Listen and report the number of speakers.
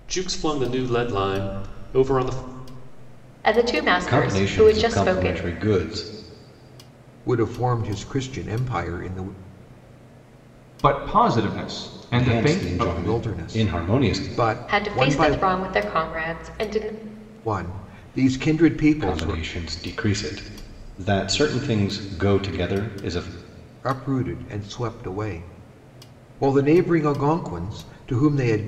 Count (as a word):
five